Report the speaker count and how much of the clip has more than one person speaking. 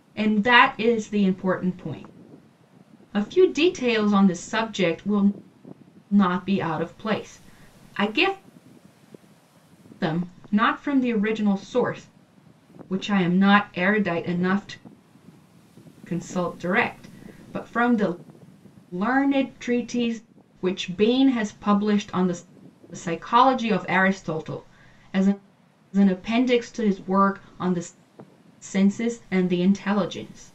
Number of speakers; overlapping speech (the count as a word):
one, no overlap